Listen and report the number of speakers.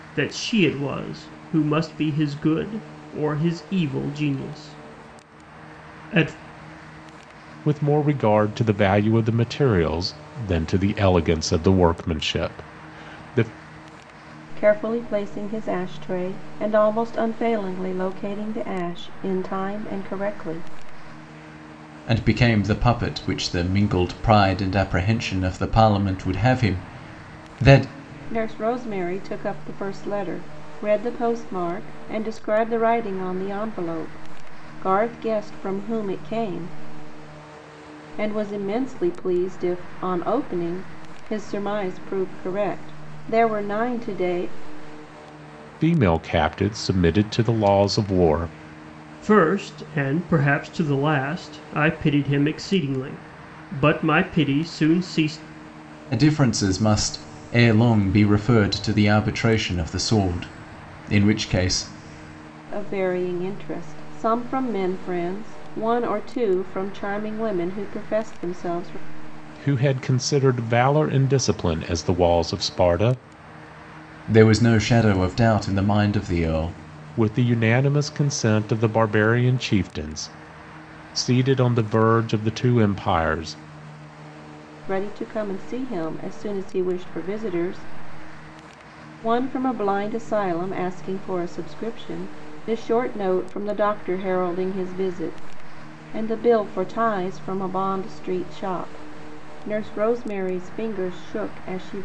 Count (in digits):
4